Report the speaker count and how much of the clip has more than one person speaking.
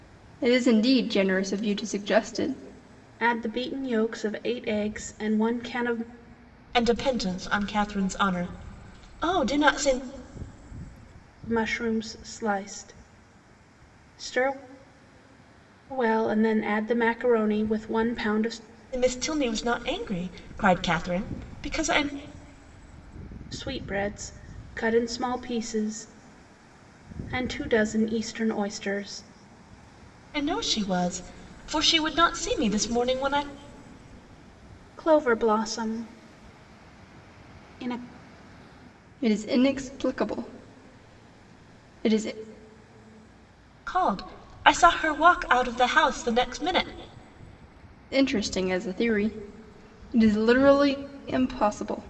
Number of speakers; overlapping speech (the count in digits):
3, no overlap